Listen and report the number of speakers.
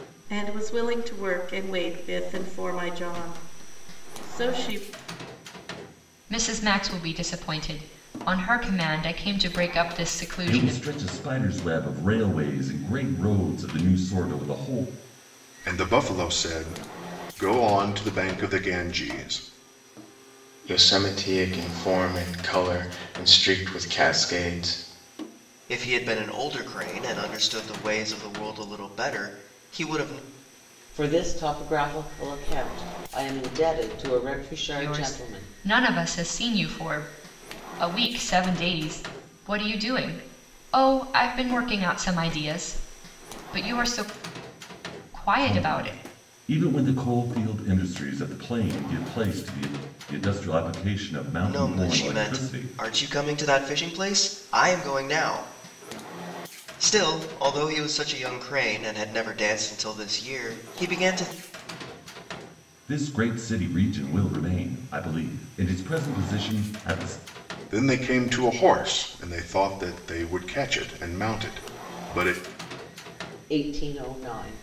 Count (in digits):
7